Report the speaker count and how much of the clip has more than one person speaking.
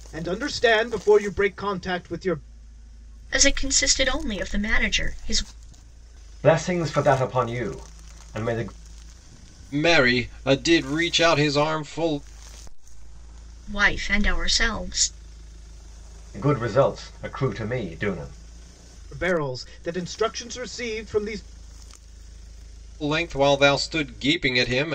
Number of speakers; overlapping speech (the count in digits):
4, no overlap